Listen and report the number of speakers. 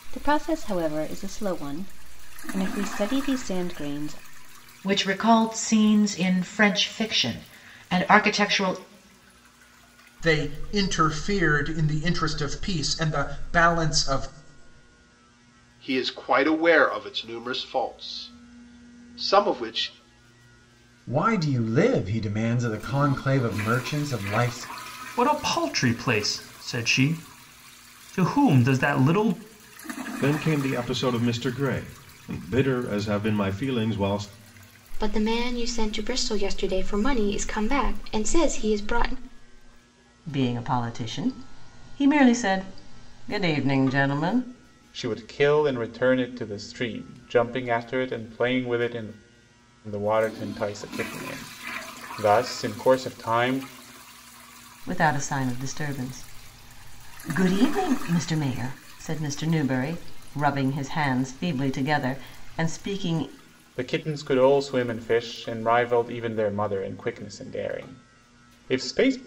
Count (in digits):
10